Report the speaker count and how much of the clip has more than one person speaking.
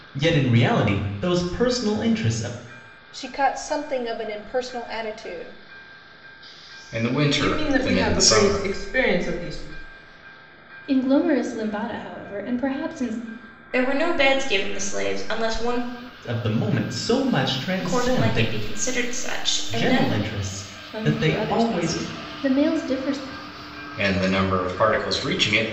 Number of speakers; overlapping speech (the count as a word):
six, about 14%